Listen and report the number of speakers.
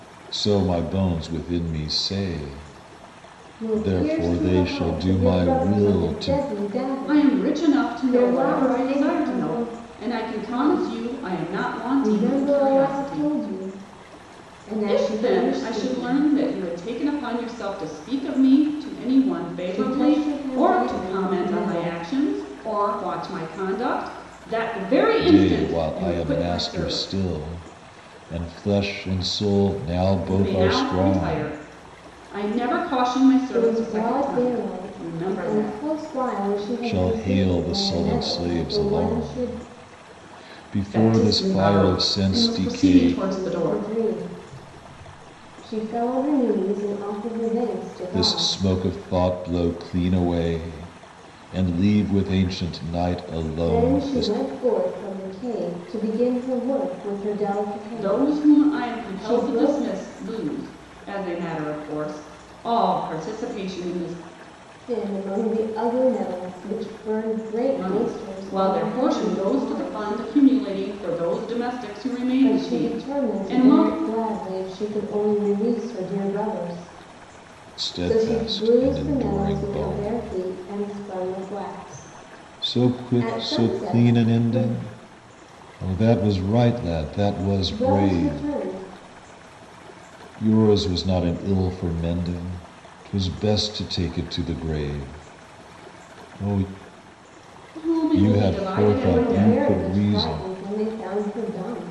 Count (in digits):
3